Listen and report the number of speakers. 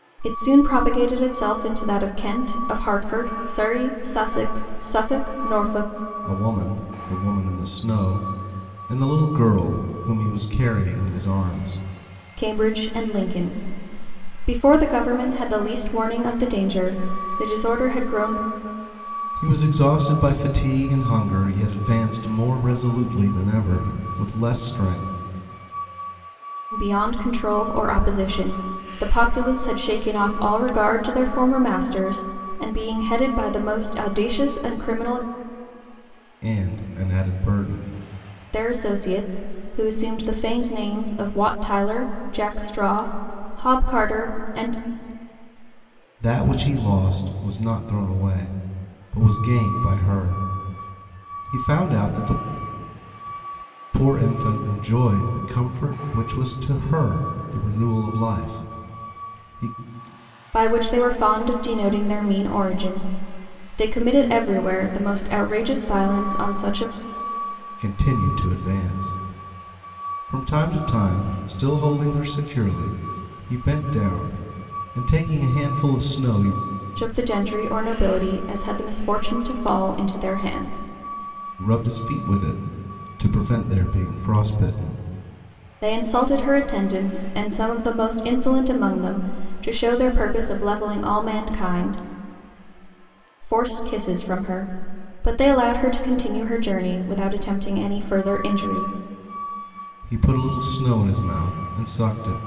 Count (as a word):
two